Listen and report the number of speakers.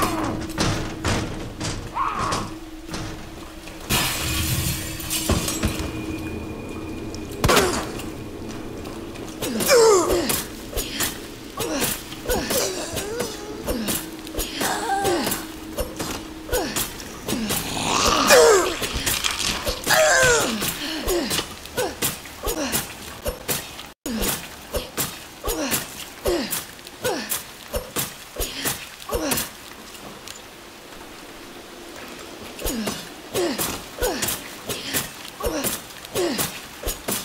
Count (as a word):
zero